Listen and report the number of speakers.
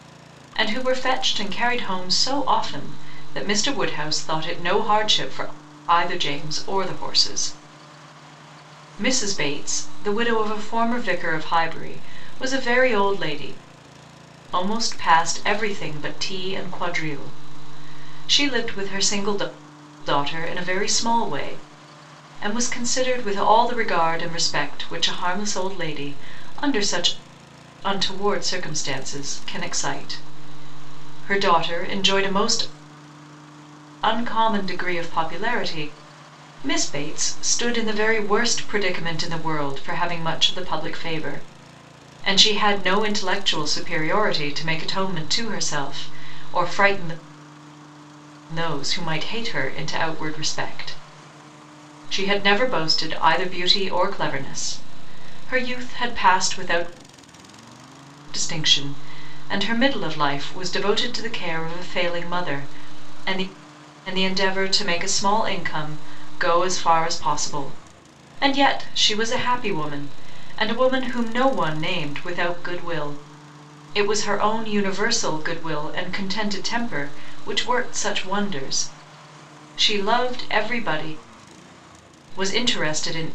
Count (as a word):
one